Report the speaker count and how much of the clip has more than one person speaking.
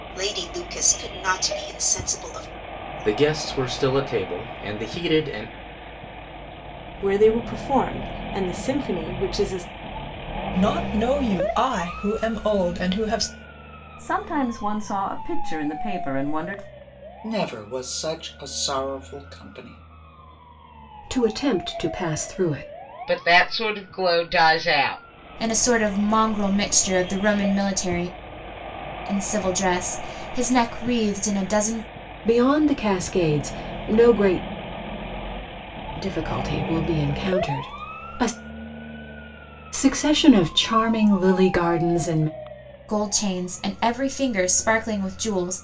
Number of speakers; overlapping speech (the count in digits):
9, no overlap